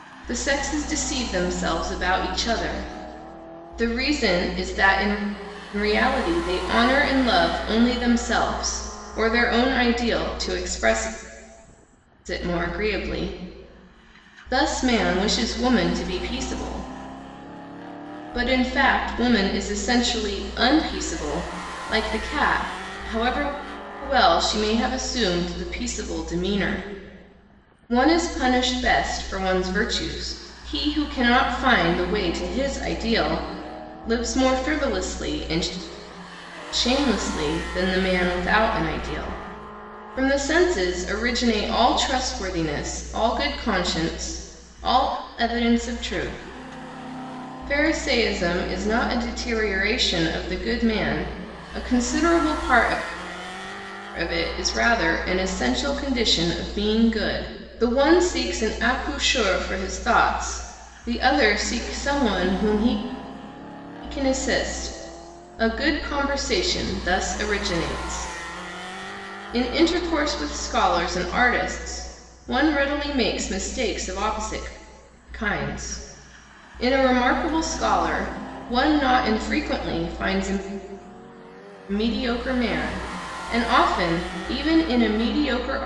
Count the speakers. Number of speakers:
one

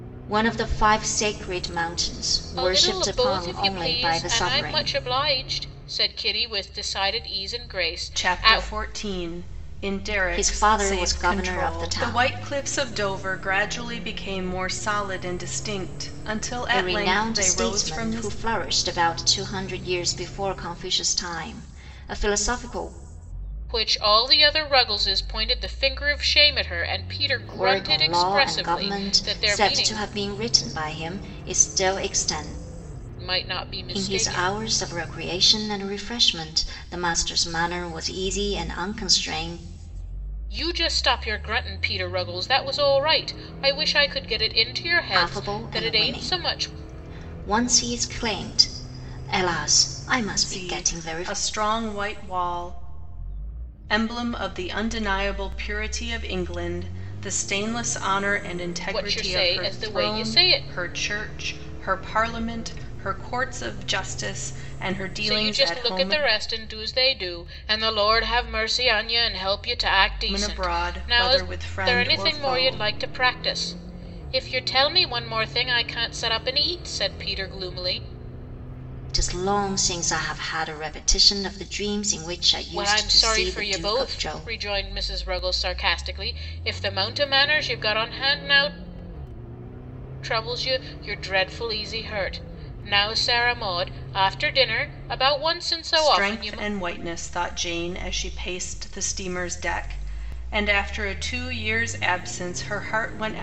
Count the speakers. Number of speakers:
three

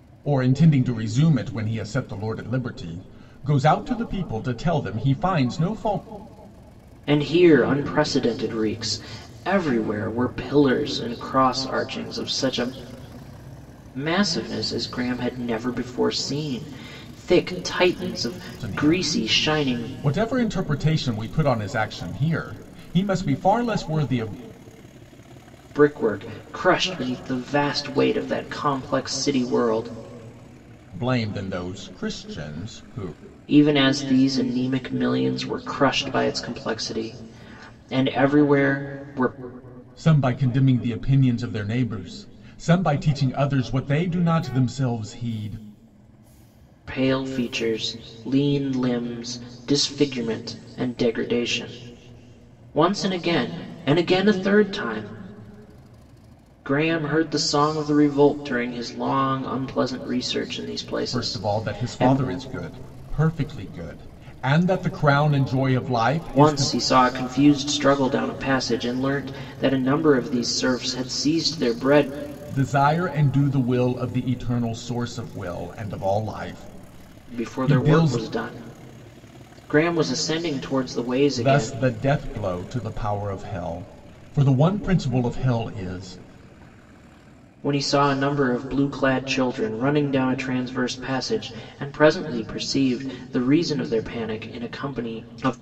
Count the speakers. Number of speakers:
two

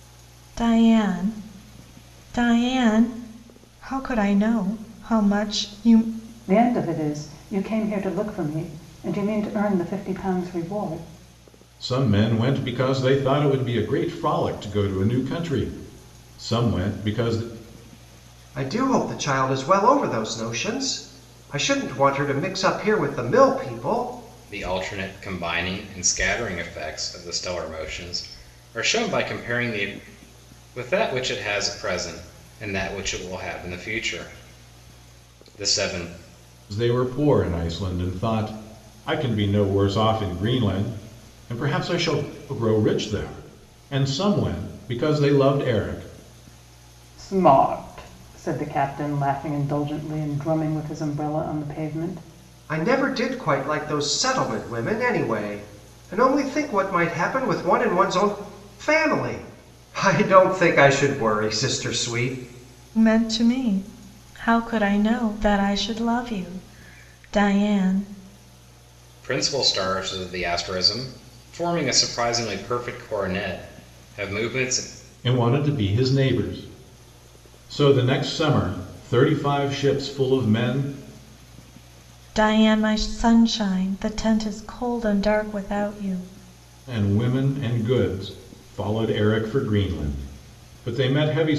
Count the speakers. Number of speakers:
five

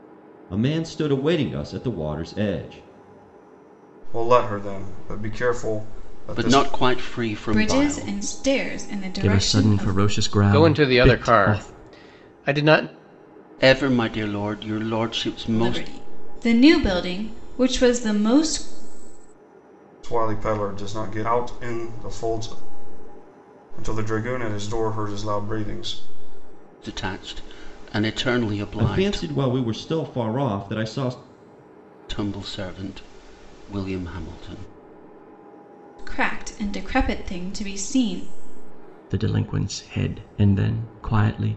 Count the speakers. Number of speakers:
six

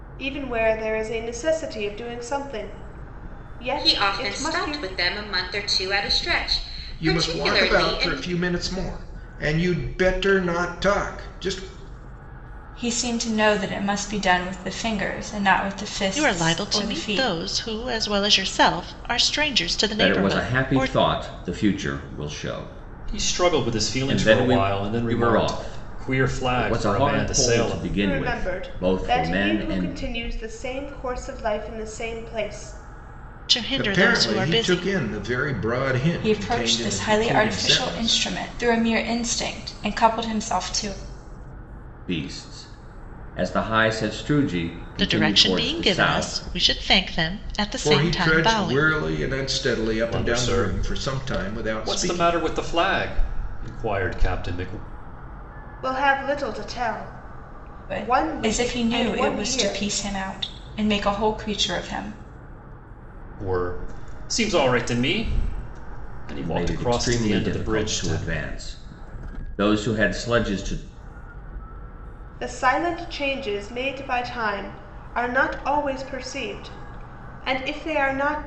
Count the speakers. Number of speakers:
seven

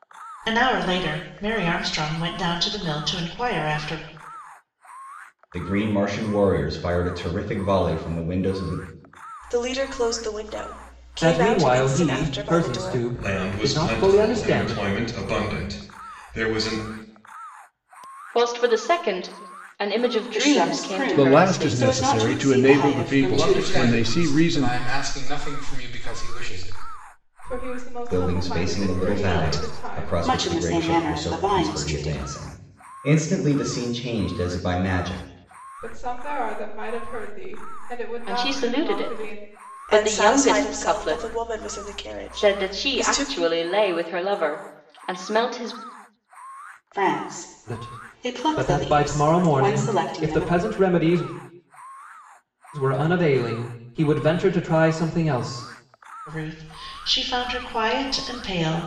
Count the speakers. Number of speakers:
ten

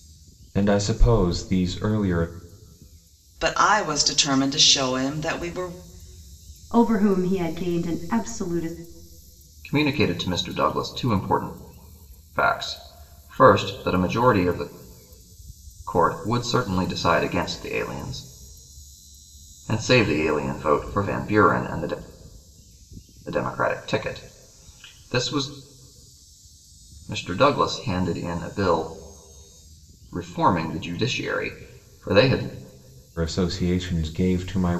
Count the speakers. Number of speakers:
four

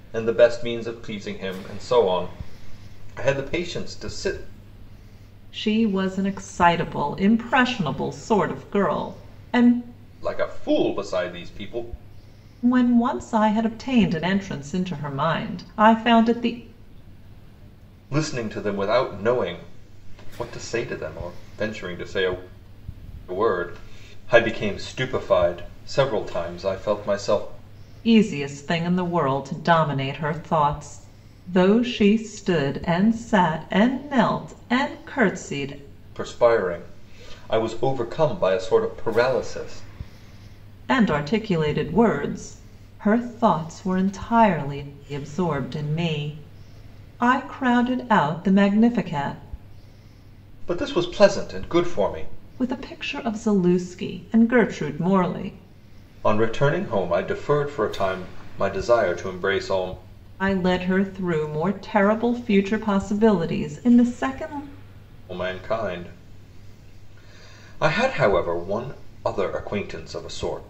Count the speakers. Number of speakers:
two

